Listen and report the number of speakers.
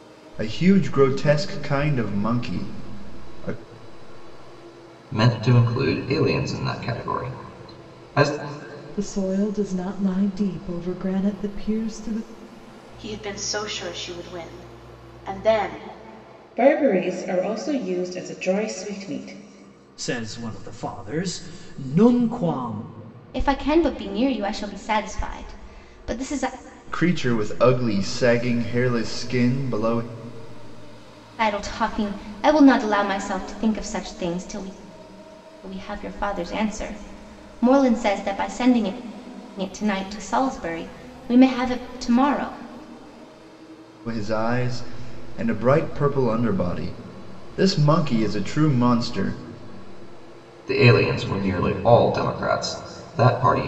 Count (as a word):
seven